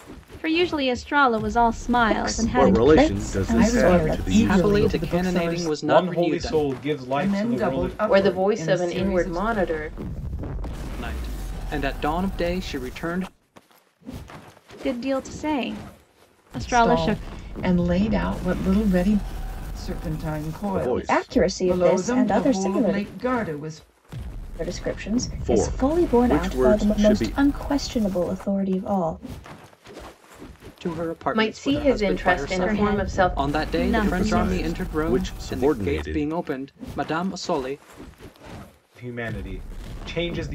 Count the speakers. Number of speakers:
eight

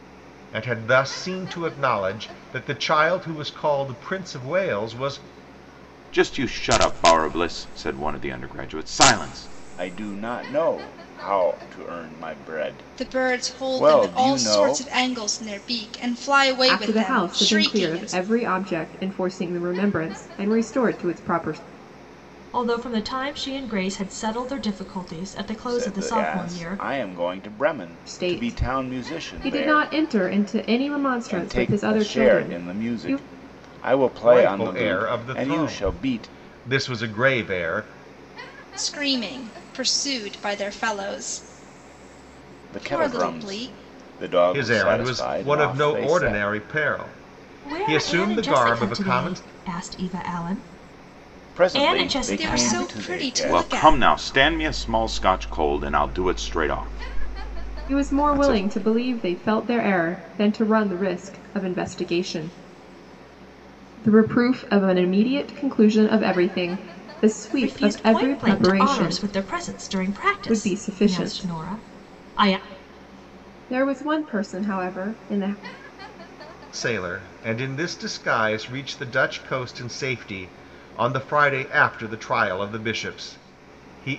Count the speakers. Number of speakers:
six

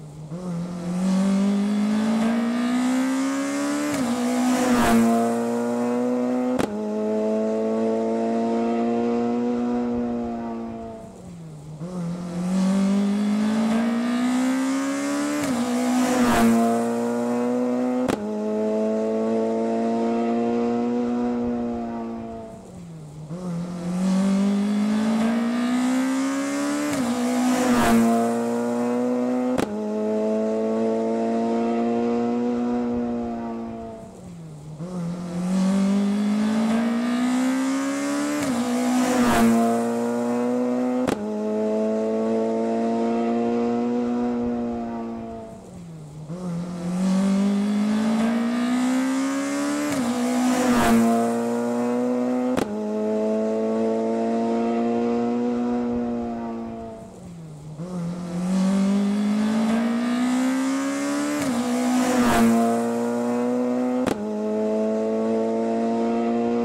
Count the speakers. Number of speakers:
zero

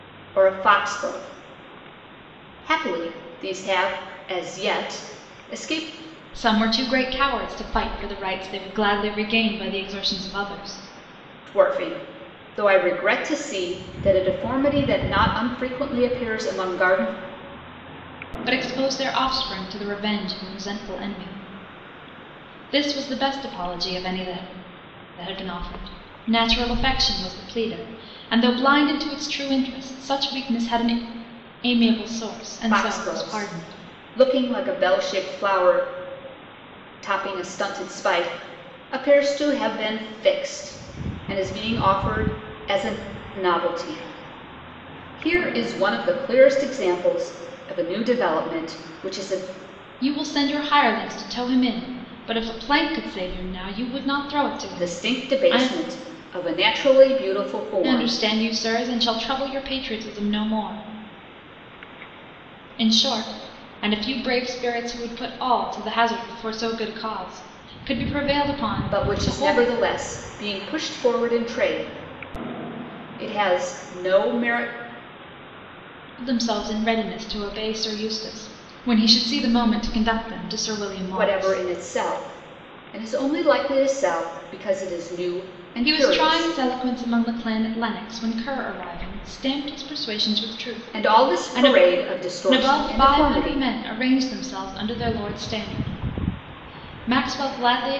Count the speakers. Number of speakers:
two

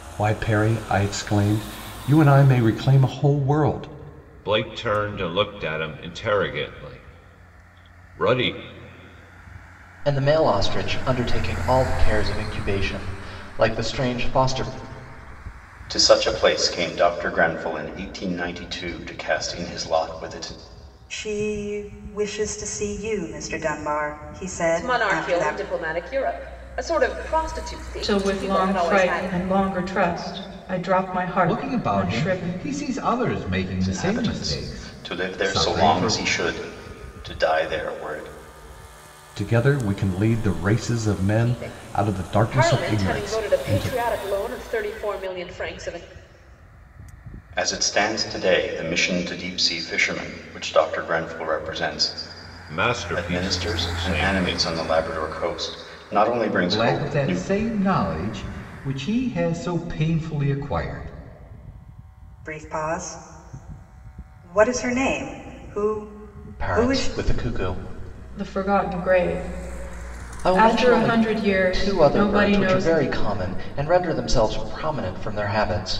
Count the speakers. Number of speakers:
eight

